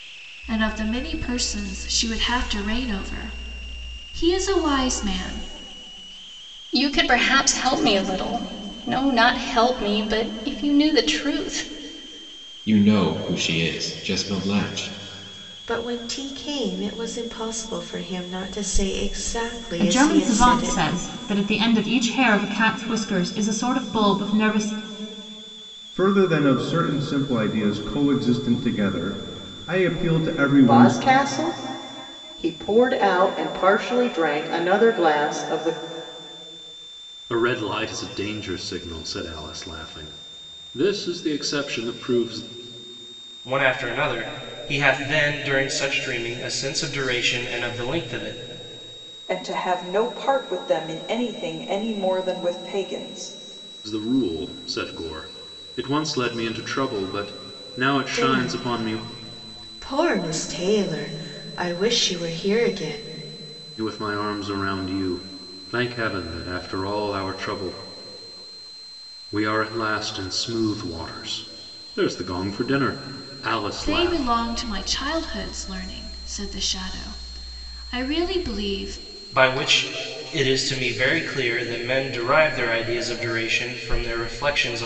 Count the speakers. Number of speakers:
10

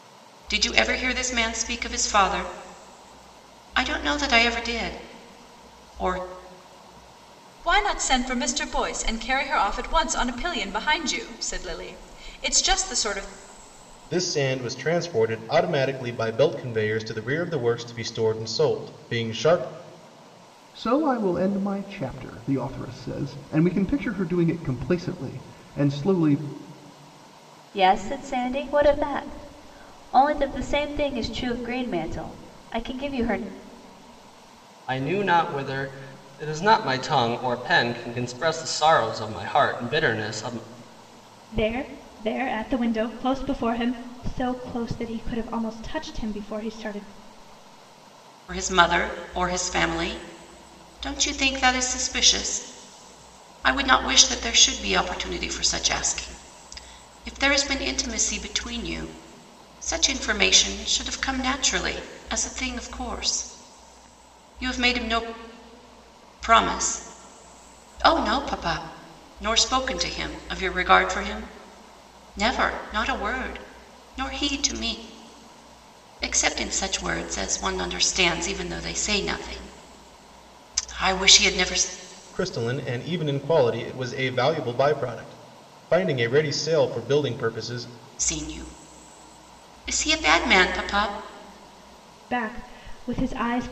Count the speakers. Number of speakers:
7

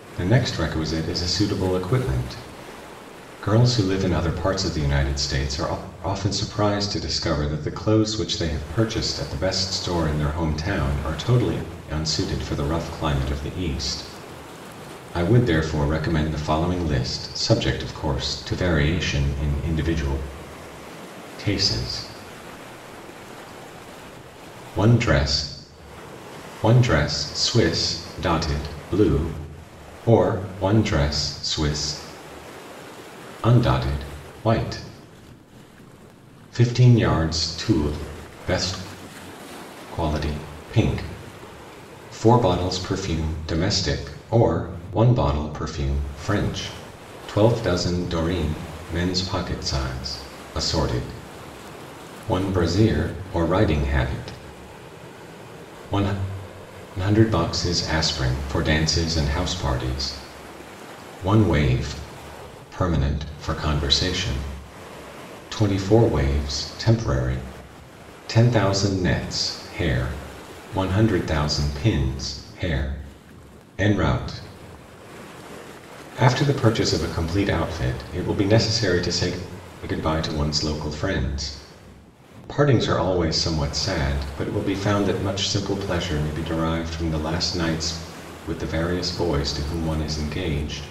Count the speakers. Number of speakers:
1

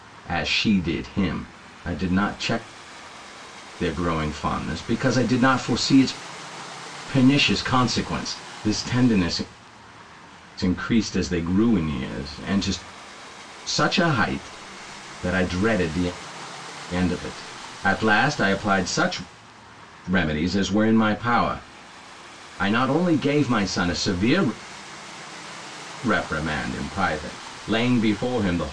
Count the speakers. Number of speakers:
1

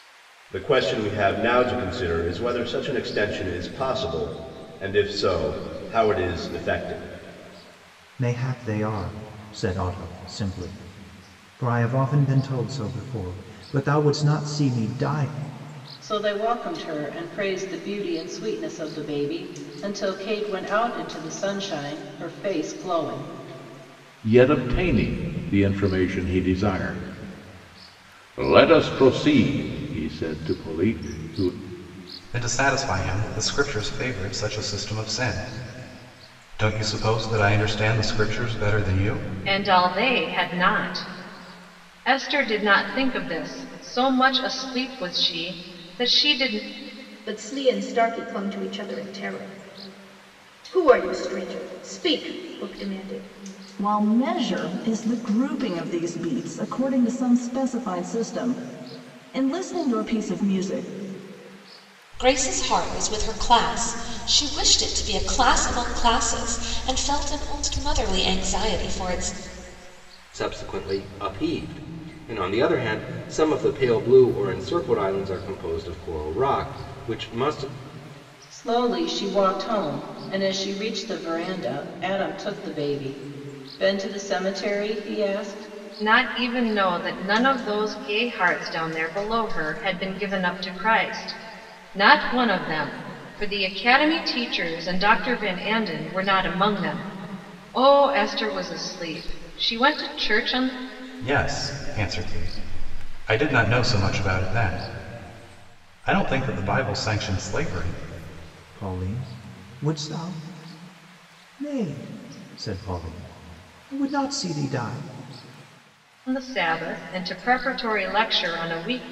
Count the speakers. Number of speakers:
10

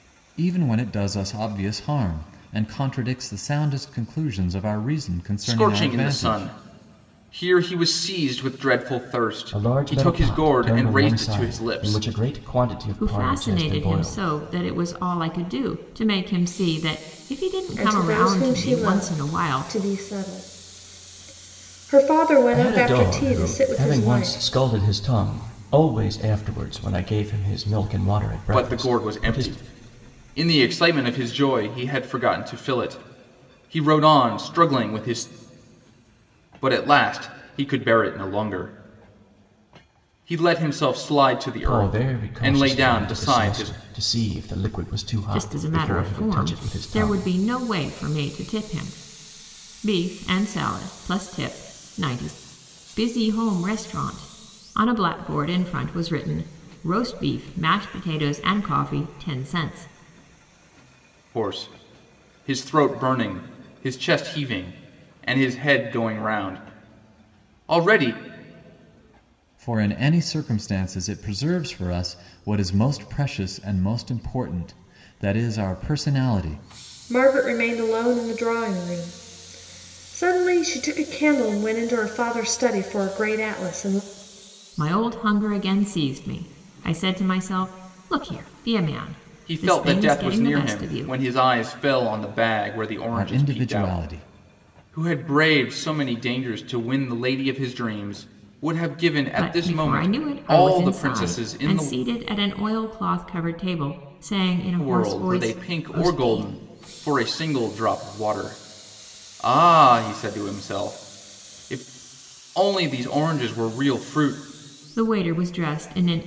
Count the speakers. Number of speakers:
5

